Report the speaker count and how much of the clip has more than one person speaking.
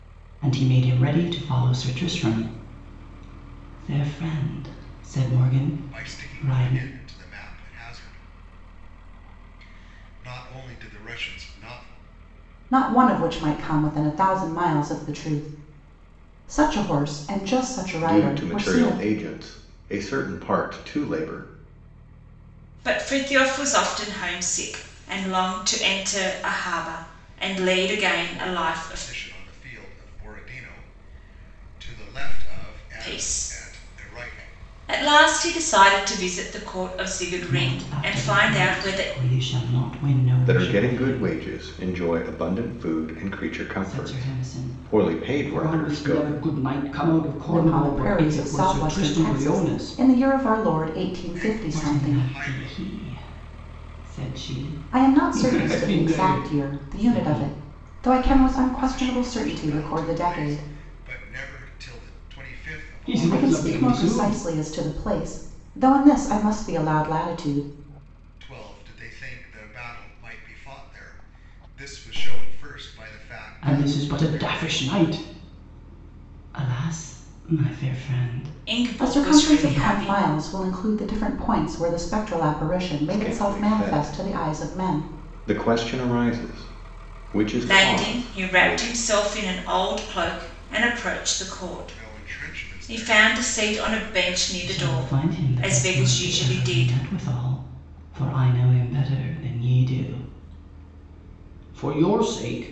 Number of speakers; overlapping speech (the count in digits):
5, about 30%